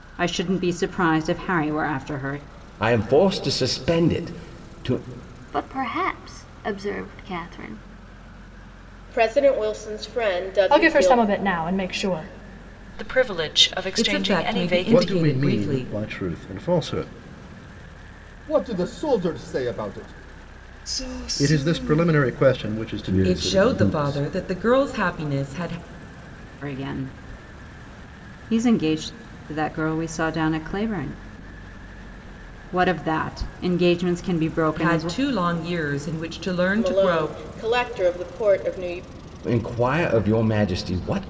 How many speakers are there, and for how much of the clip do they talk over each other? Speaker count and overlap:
ten, about 13%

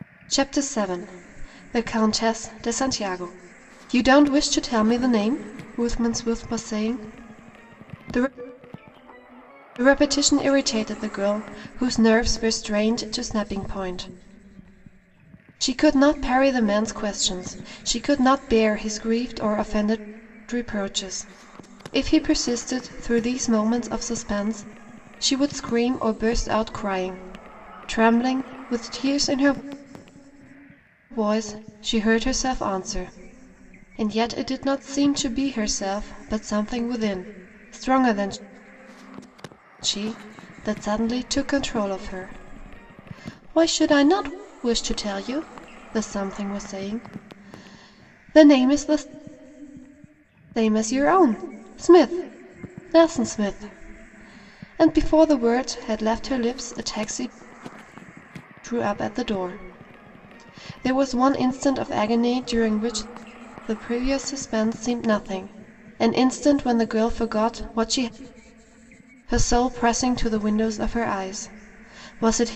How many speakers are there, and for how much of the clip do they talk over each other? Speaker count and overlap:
one, no overlap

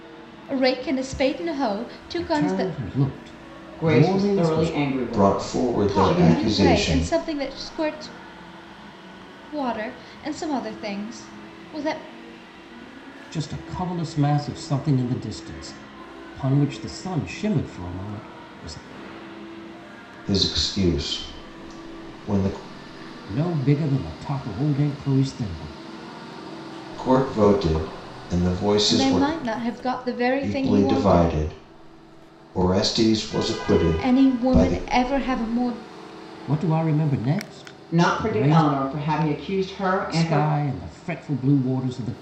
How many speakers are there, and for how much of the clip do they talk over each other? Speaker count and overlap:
four, about 18%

